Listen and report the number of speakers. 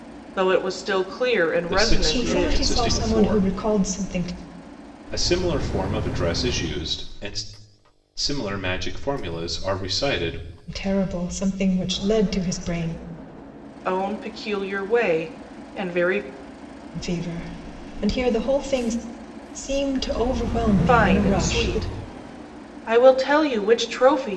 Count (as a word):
three